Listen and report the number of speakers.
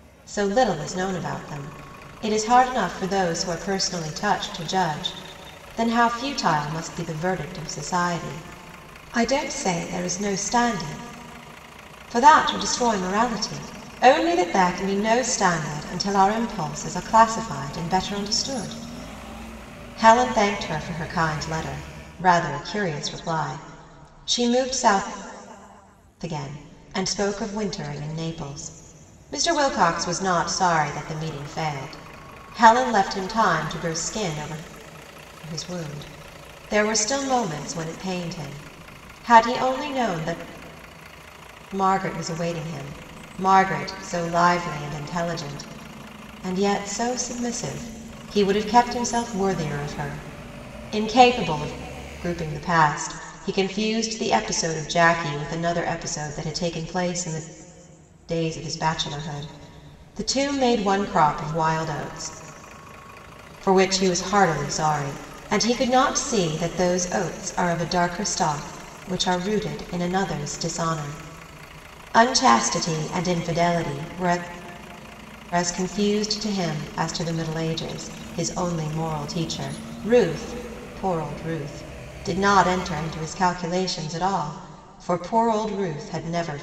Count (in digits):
1